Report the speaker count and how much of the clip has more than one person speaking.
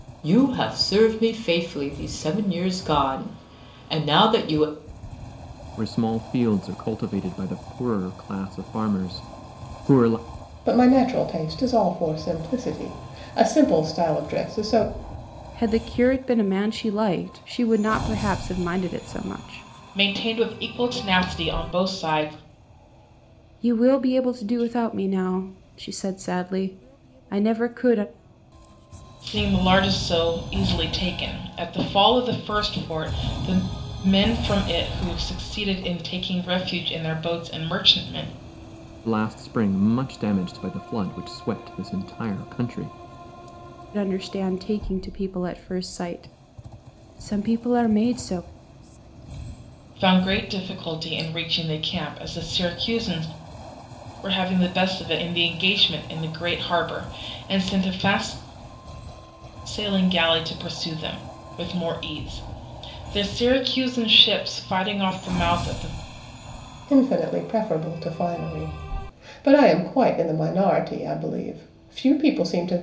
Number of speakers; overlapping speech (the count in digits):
5, no overlap